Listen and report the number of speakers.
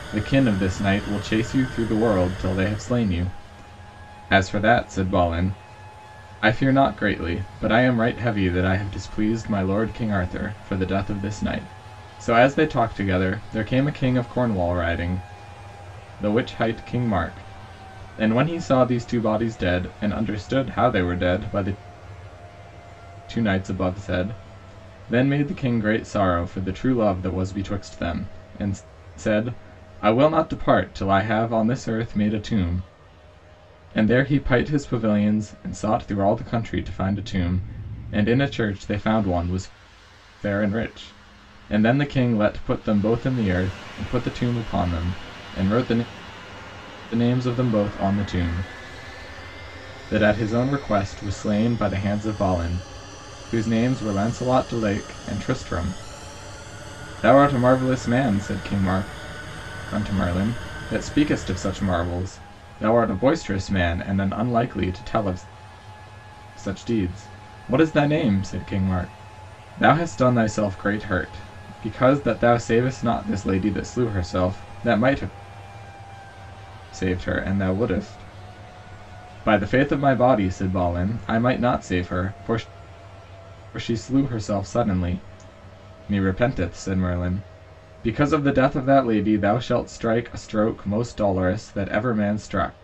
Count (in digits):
1